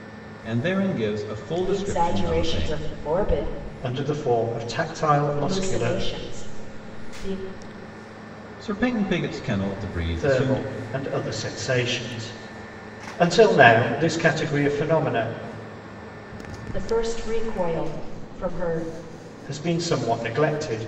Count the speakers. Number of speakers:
three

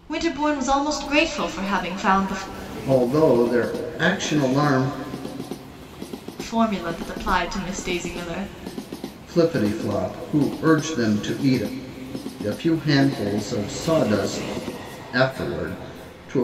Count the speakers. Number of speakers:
two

